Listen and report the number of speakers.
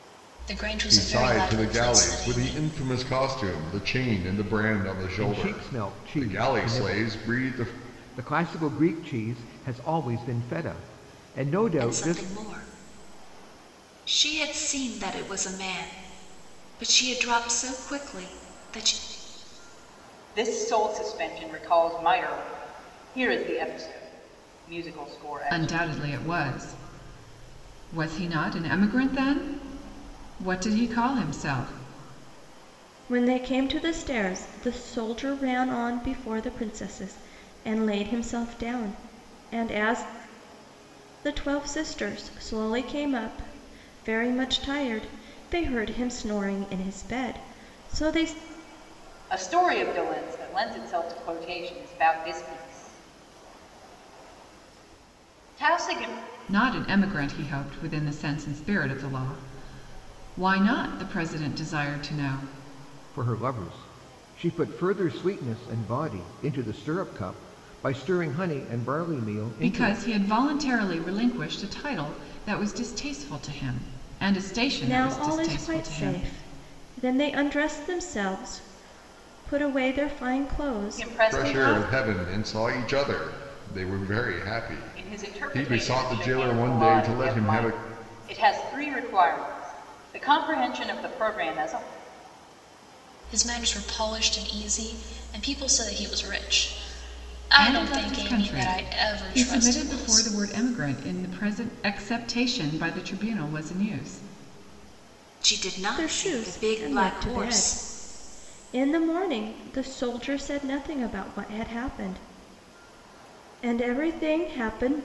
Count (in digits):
7